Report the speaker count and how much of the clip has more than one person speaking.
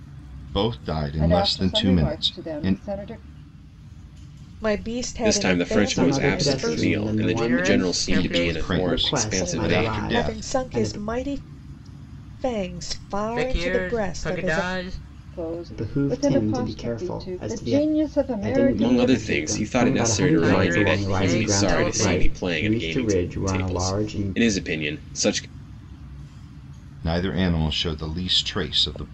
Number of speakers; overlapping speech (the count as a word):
six, about 58%